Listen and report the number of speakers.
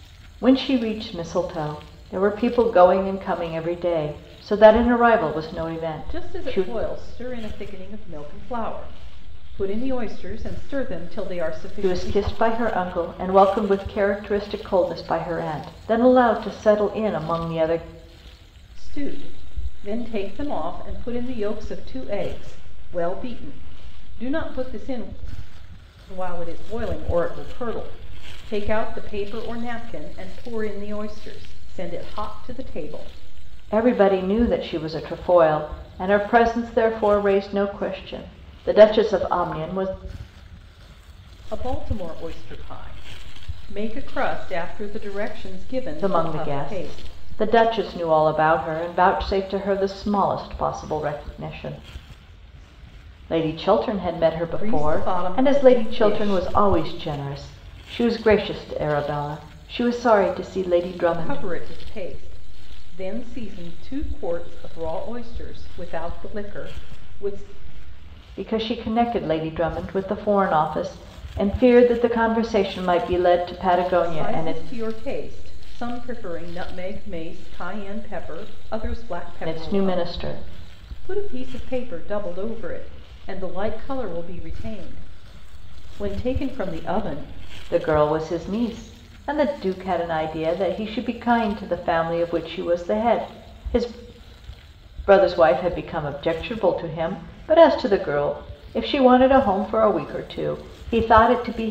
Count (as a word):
two